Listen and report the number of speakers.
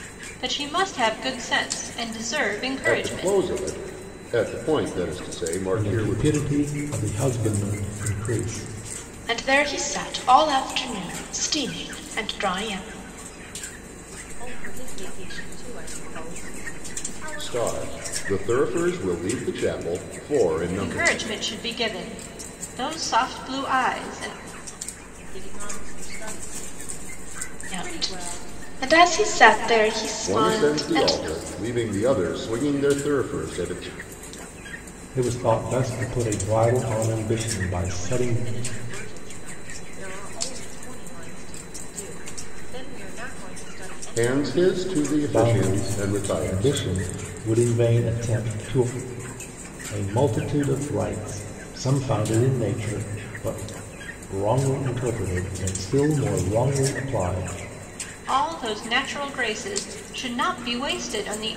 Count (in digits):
5